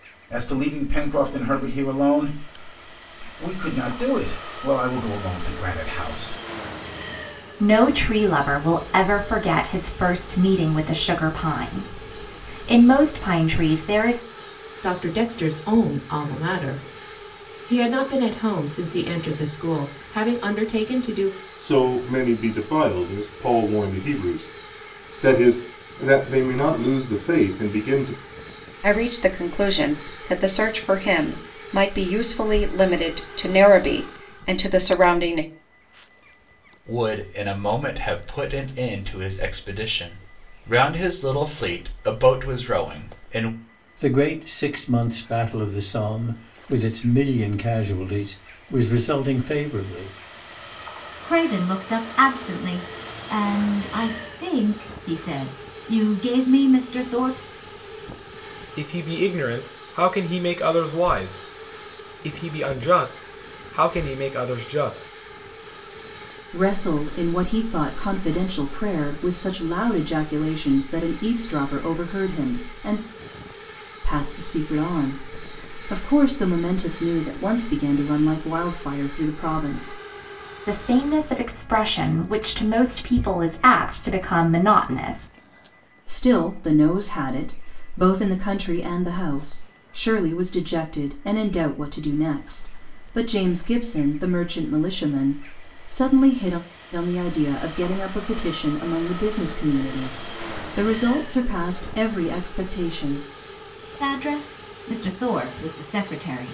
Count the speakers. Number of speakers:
10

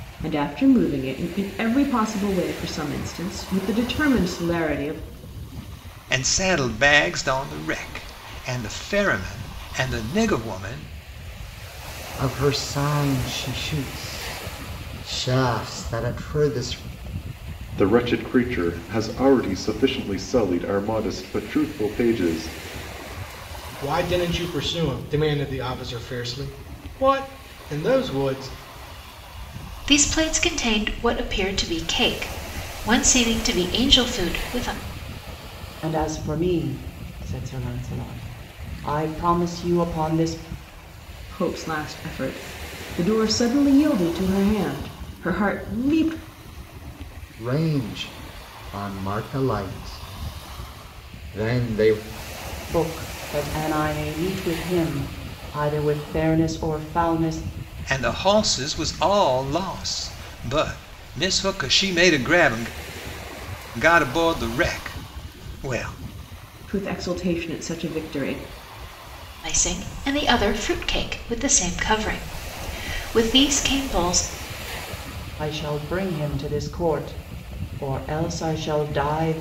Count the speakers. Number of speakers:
7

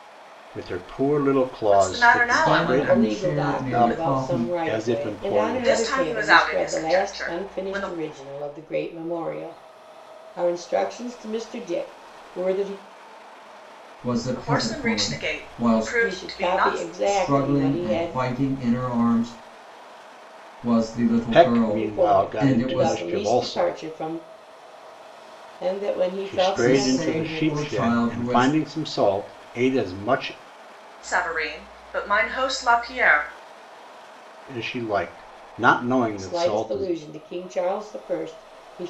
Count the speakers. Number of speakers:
4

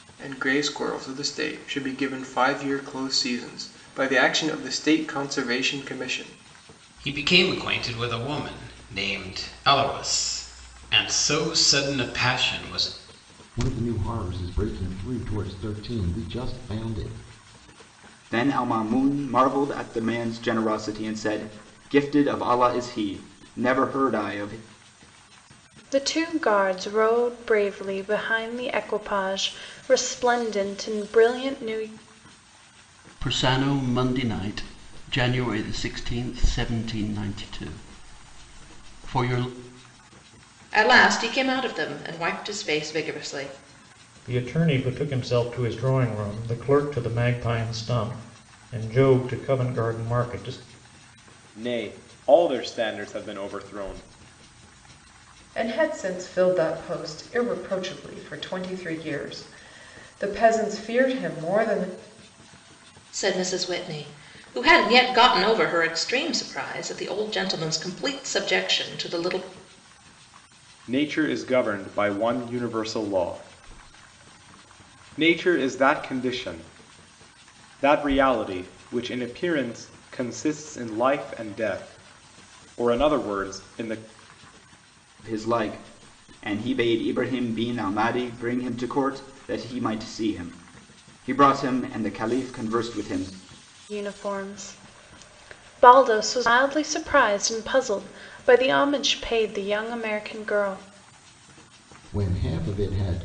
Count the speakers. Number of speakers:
10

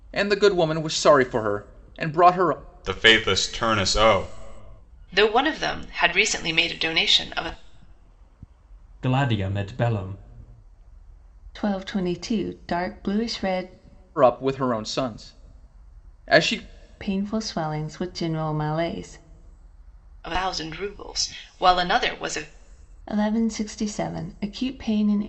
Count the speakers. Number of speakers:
5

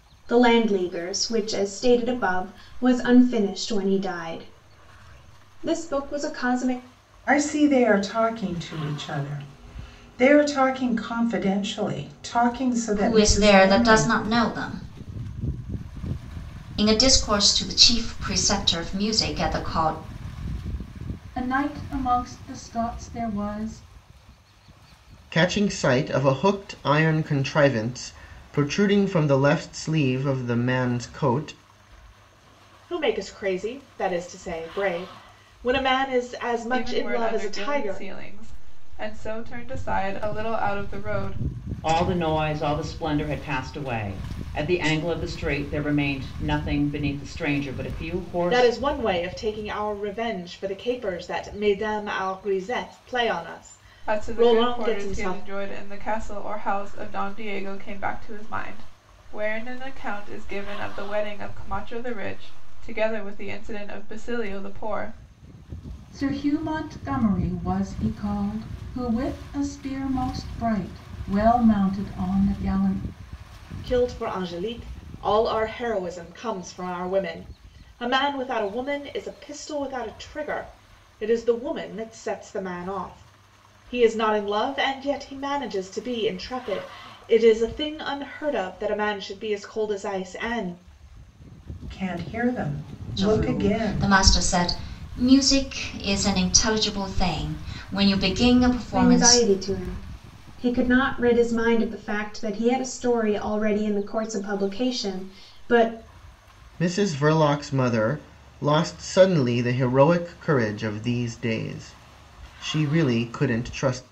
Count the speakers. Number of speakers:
8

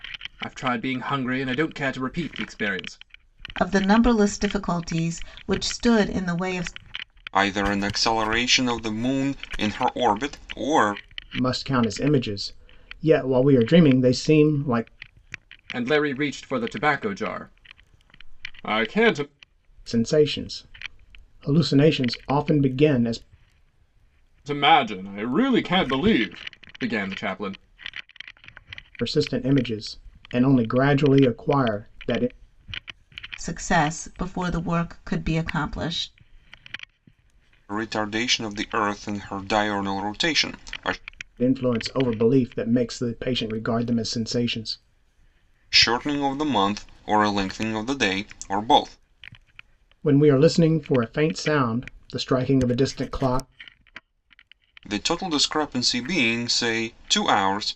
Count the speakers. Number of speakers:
4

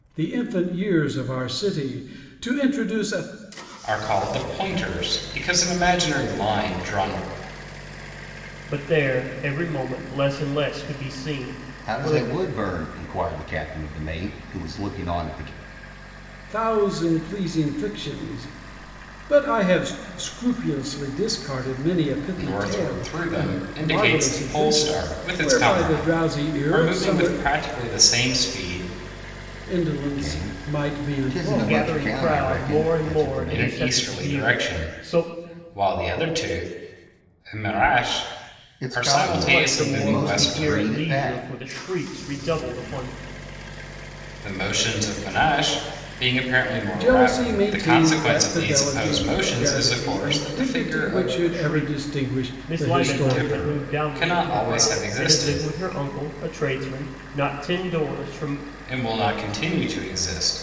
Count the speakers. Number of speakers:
4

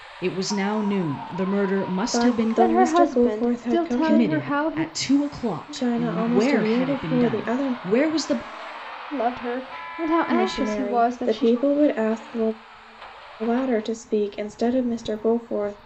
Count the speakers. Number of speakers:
3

